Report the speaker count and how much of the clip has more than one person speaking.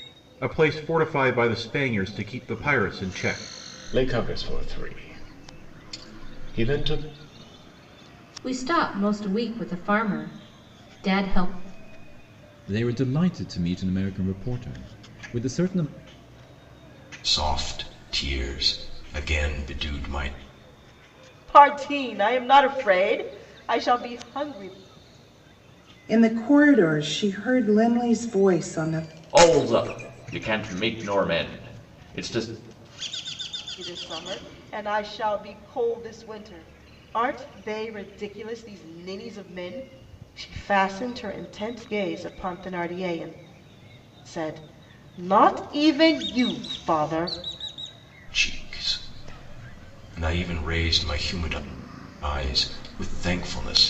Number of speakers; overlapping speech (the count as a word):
eight, no overlap